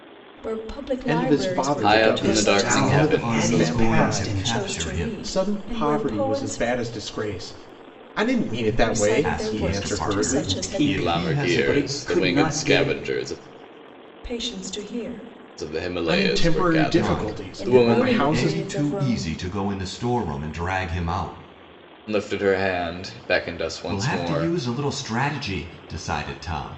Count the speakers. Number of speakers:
five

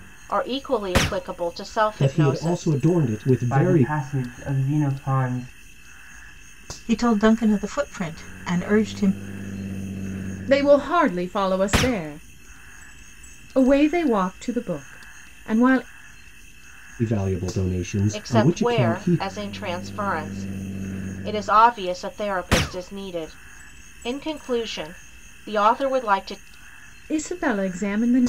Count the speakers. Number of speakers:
five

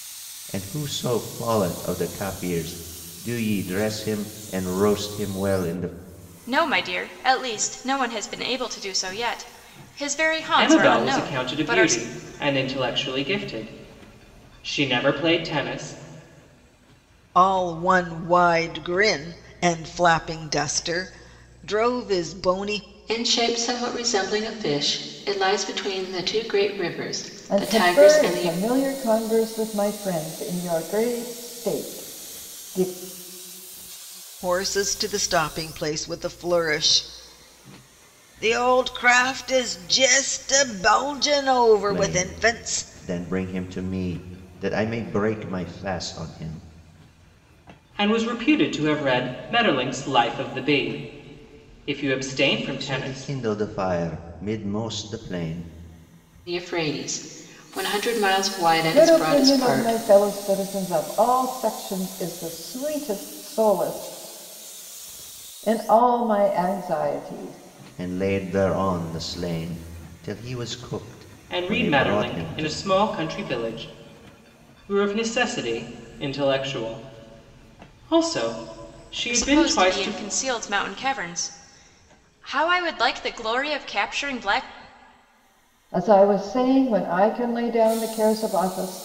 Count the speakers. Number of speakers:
six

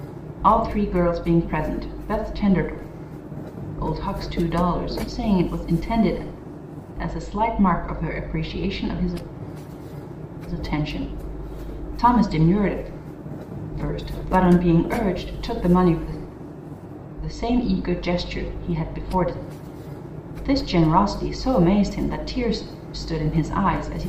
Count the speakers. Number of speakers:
one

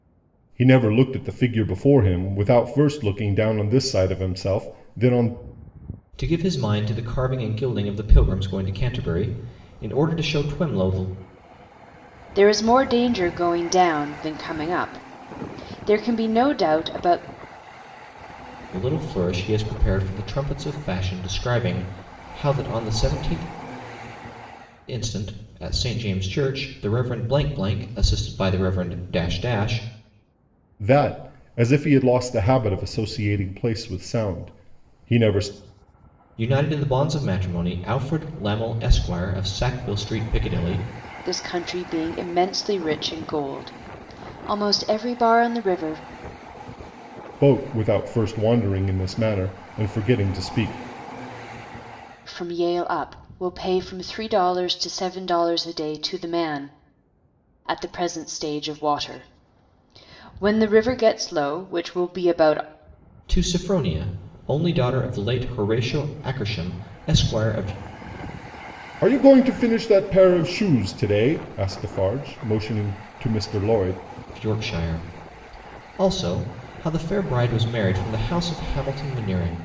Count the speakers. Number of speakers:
three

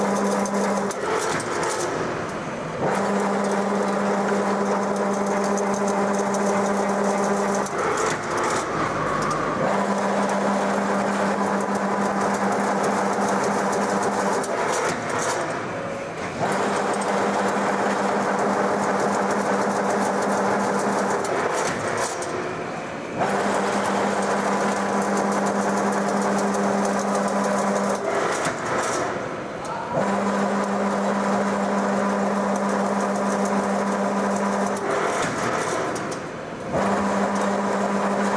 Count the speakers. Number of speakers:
zero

